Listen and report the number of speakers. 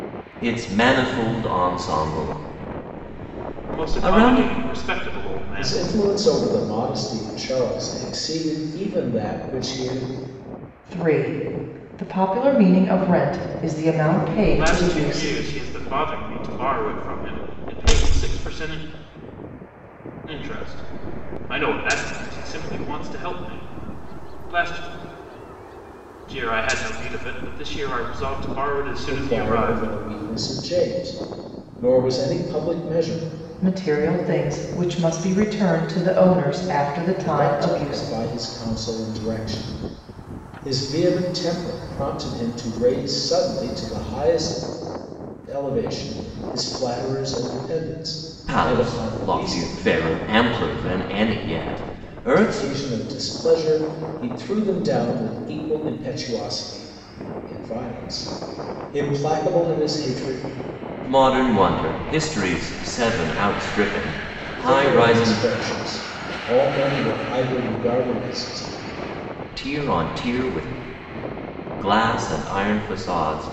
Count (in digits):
4